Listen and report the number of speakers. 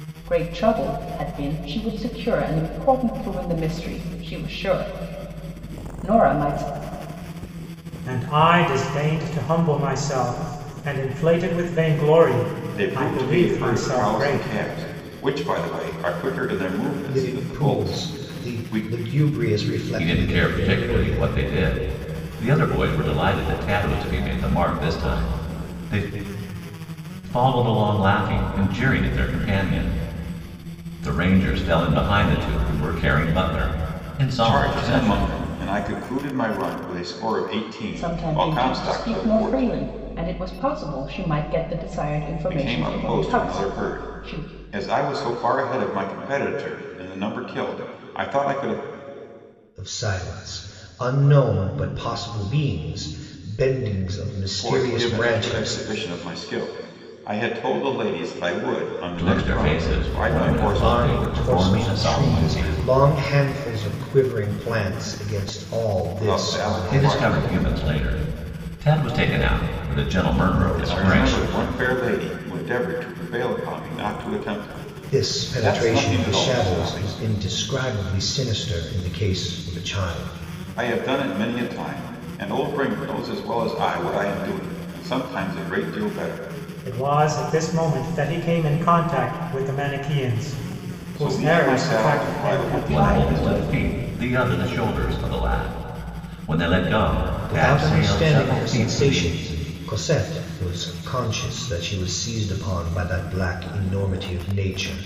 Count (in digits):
5